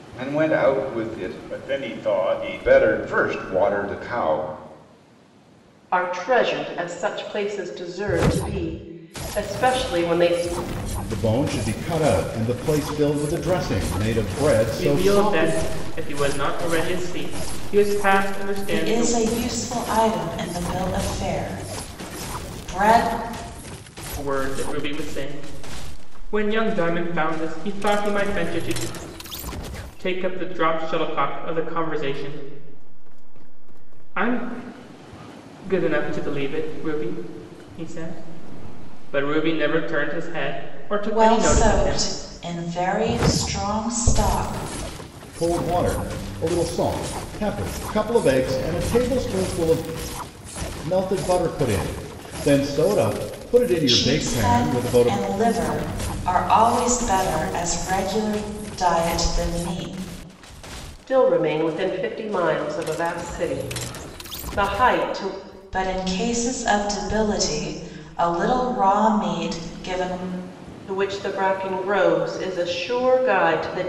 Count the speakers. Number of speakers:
5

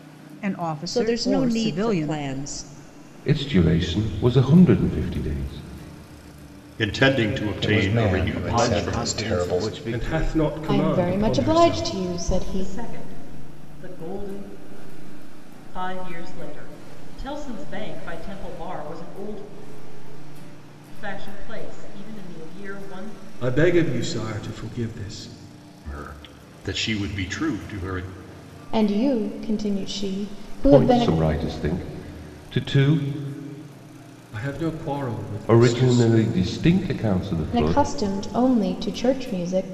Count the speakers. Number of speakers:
9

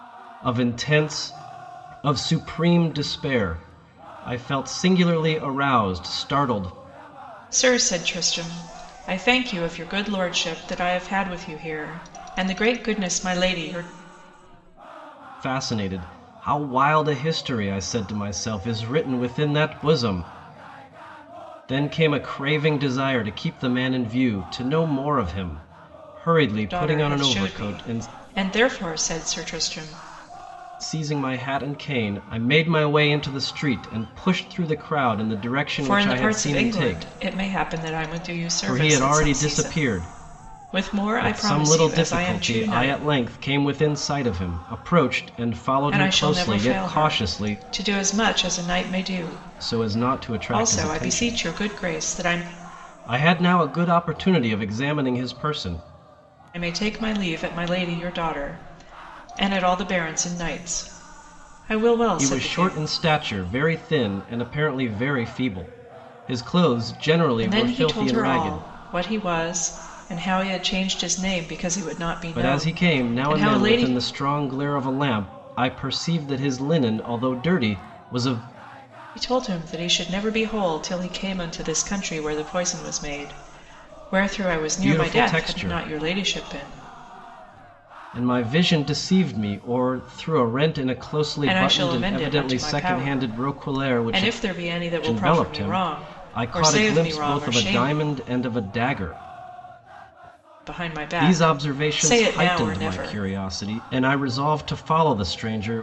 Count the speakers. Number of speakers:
2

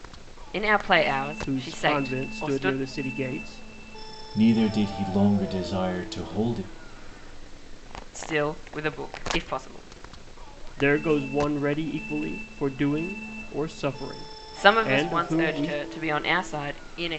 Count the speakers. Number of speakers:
3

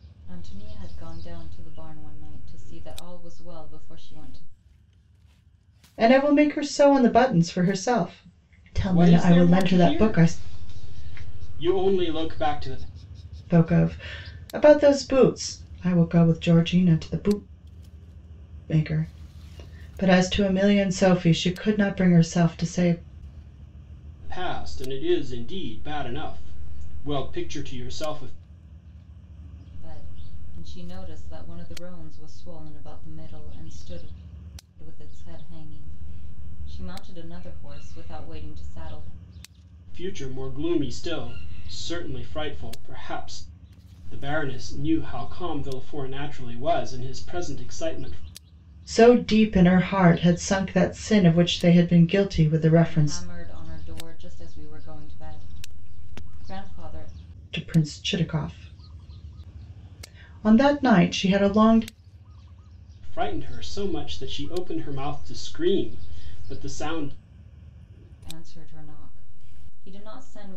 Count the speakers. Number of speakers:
3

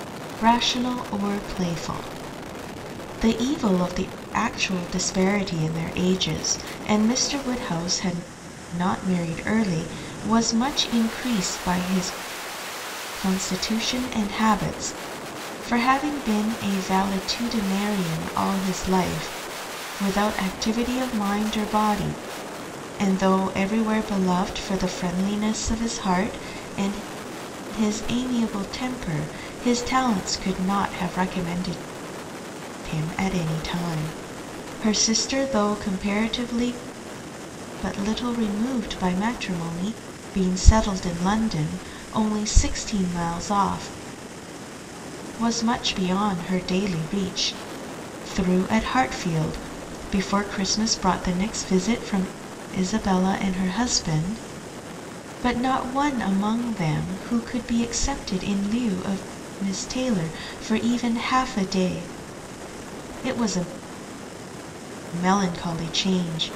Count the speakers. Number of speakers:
1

